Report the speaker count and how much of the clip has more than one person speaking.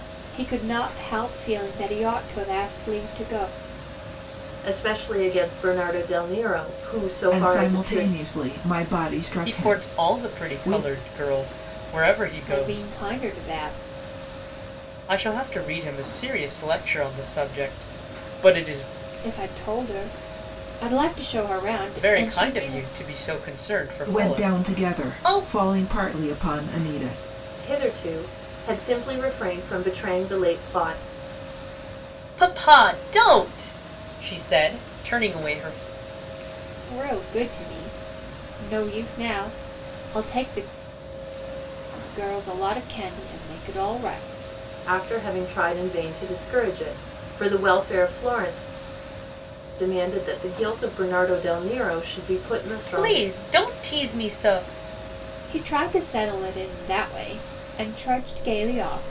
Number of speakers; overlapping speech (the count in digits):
4, about 10%